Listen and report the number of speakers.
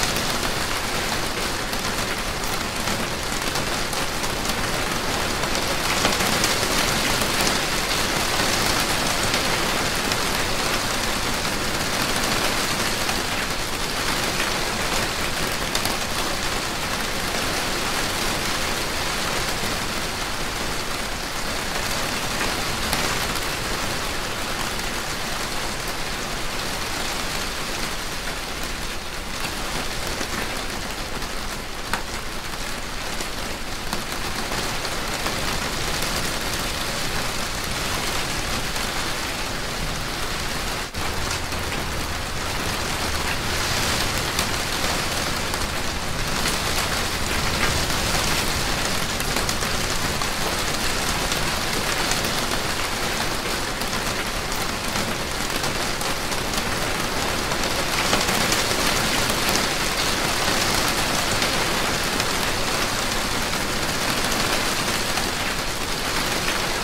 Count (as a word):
zero